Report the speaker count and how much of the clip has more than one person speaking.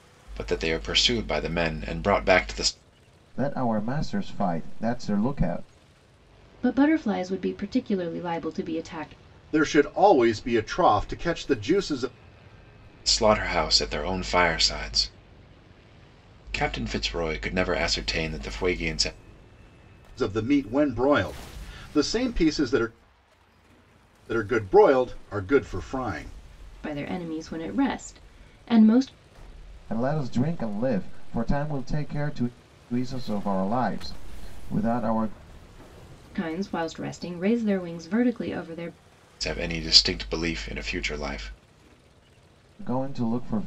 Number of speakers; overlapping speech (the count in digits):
4, no overlap